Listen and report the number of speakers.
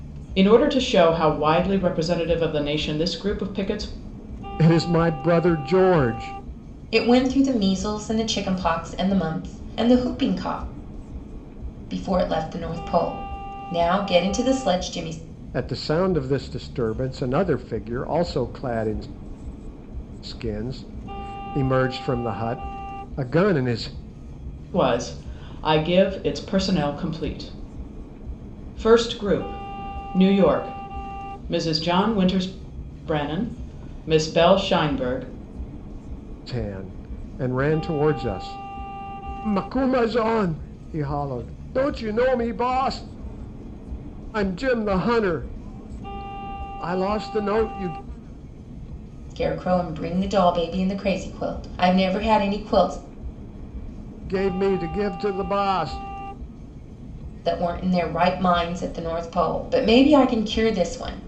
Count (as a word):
three